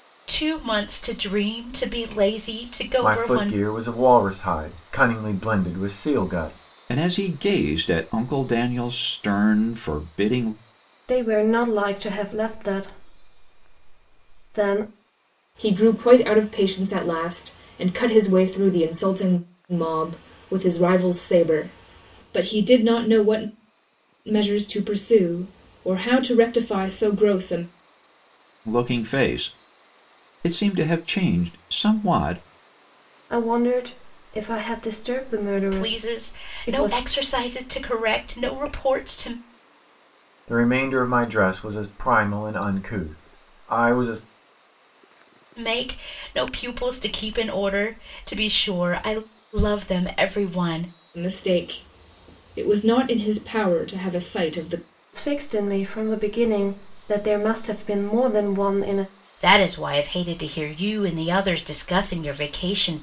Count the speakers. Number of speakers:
5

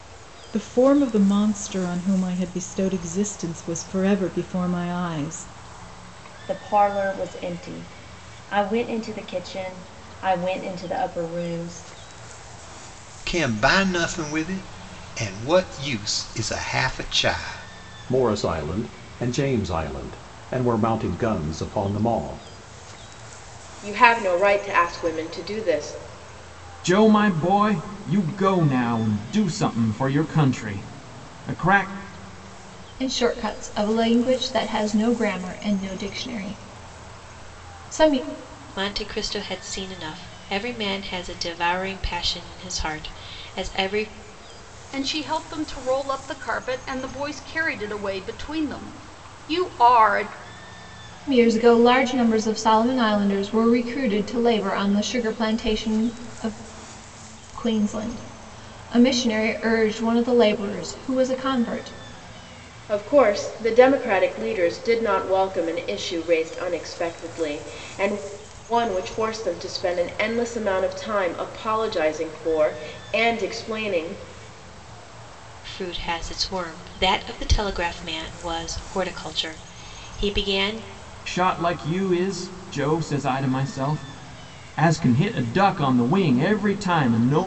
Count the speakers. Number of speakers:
9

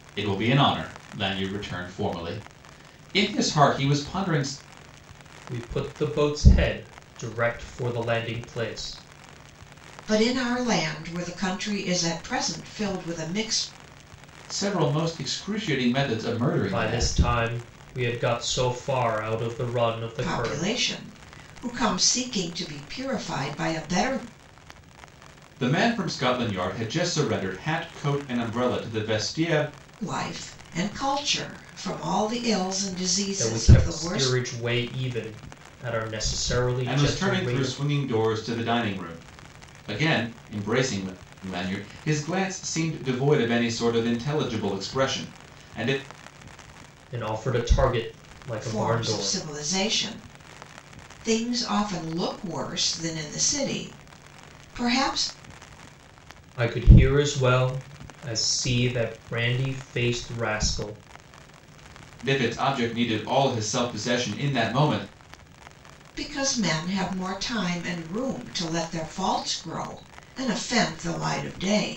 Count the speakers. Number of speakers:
3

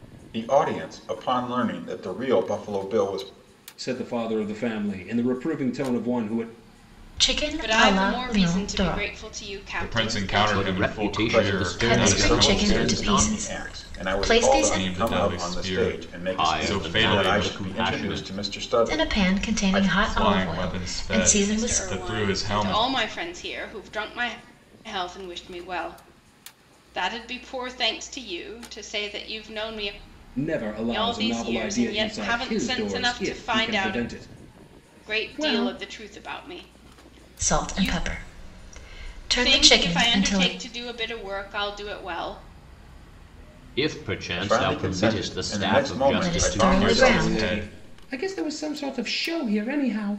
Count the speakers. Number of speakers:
6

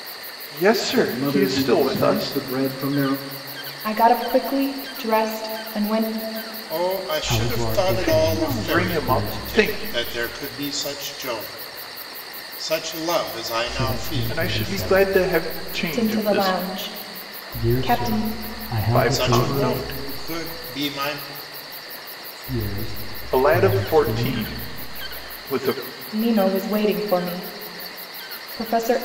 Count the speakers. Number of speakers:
5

